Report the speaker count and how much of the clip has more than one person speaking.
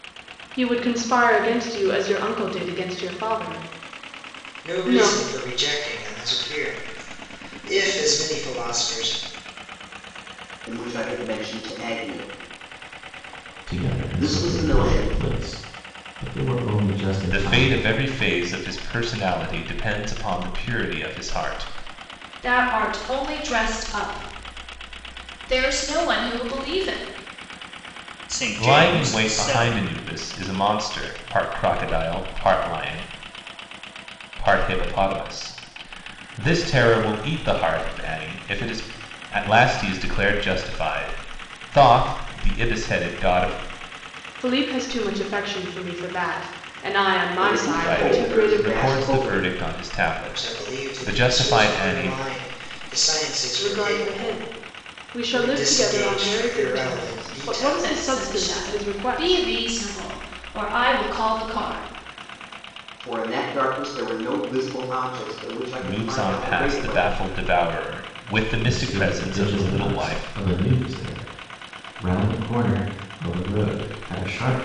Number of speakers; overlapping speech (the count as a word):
seven, about 21%